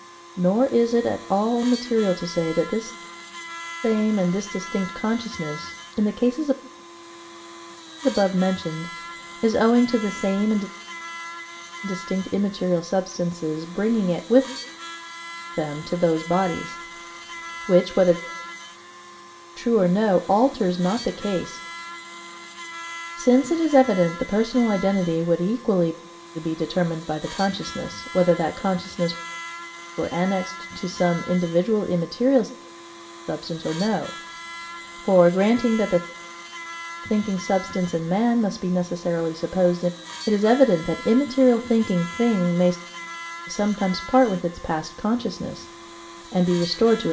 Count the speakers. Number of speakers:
1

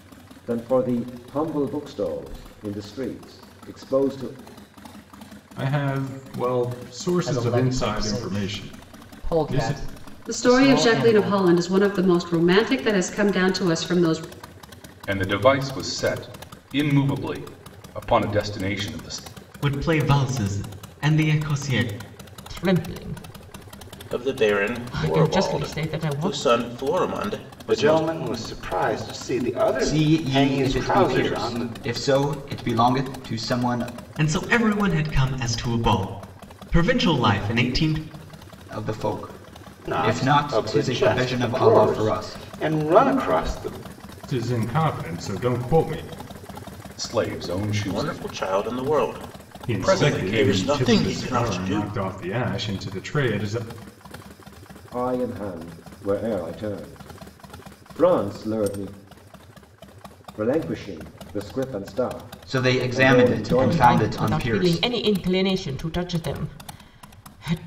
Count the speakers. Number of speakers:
10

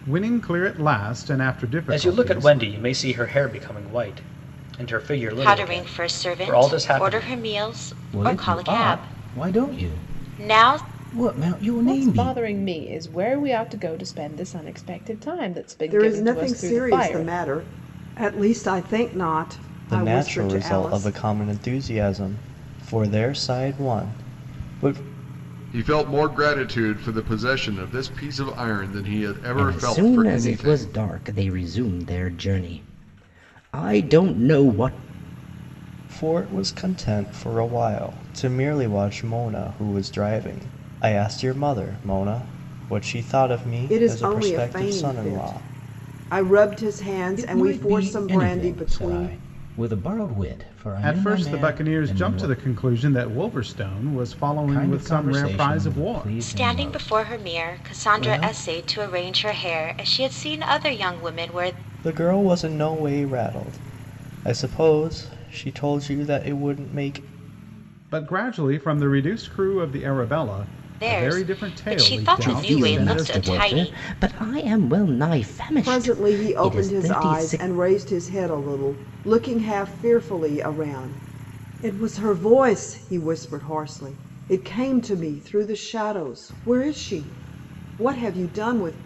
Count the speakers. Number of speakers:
9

